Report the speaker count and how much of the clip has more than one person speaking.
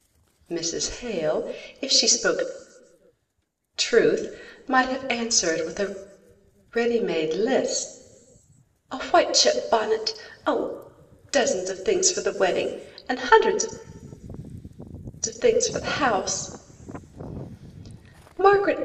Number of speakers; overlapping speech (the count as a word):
one, no overlap